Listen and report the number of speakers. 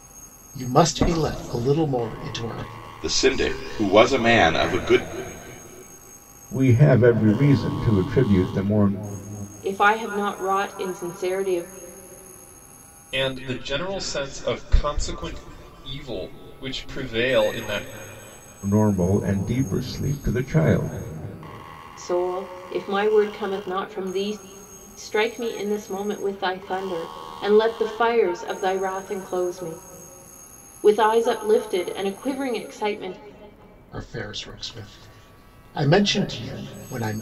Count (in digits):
5